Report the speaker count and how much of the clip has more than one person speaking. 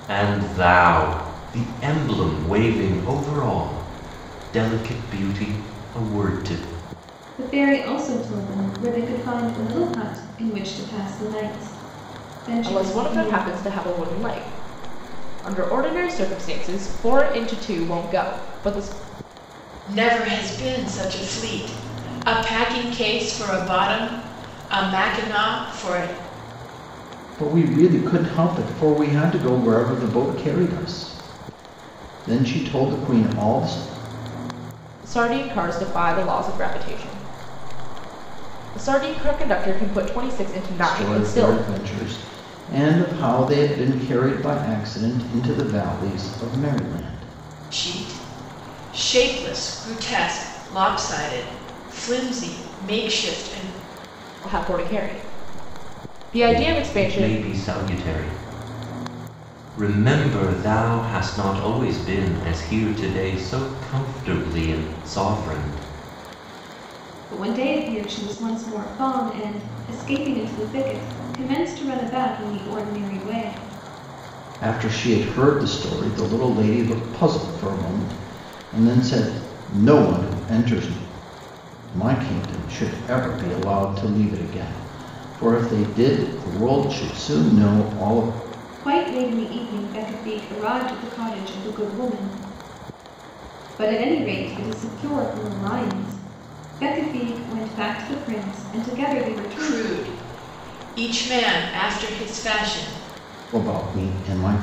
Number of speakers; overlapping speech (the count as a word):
five, about 3%